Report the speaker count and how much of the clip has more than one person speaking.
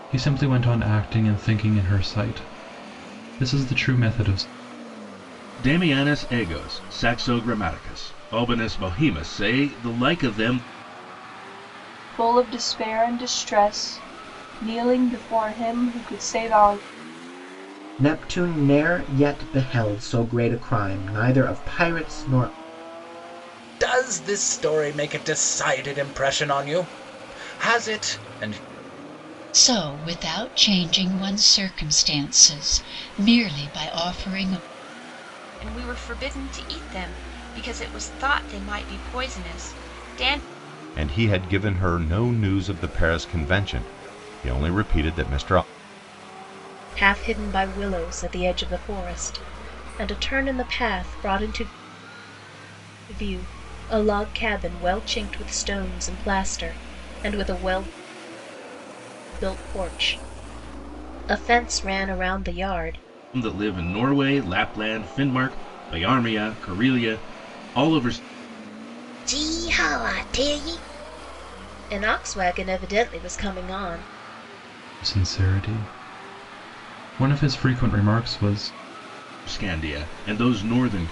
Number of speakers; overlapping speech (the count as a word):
nine, no overlap